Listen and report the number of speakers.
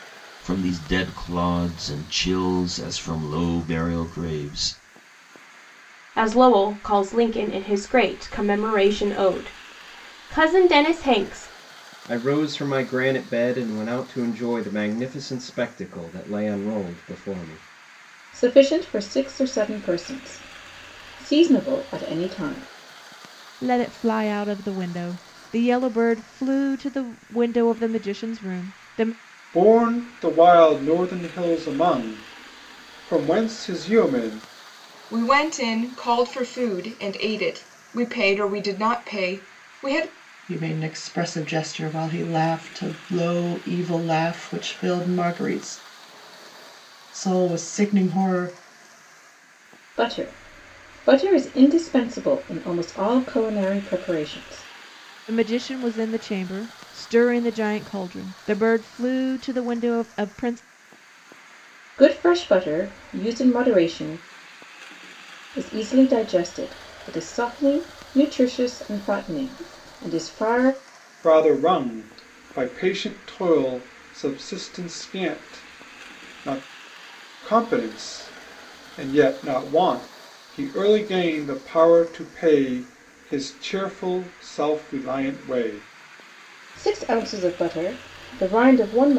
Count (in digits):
8